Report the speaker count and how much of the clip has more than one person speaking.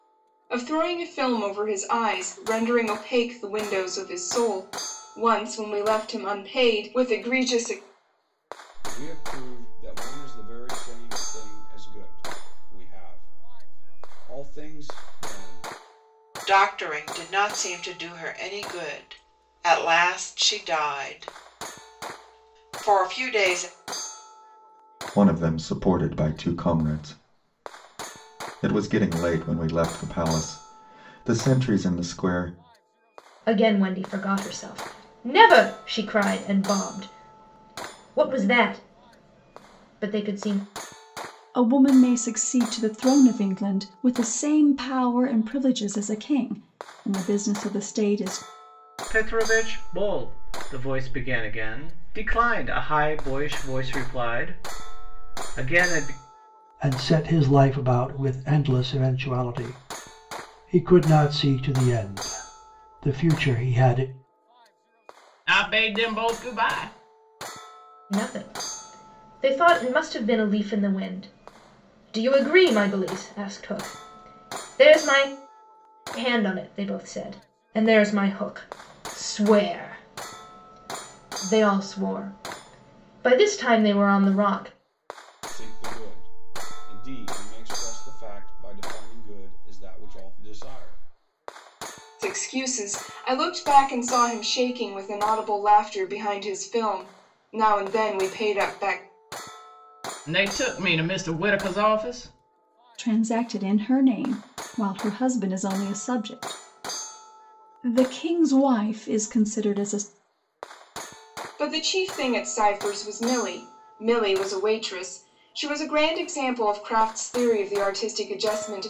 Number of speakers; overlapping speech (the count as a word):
nine, no overlap